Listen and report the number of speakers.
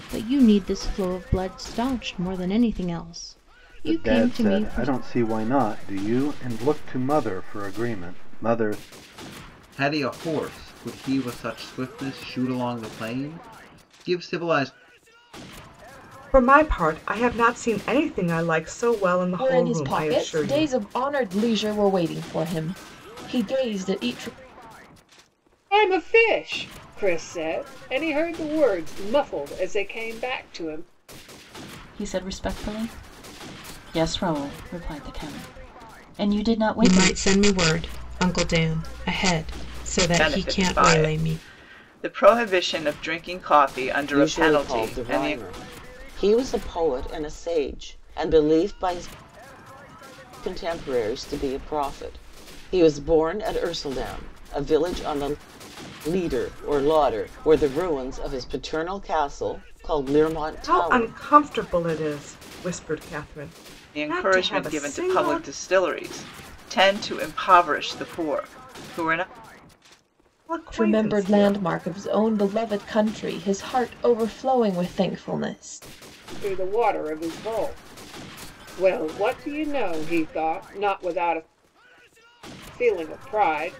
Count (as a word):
ten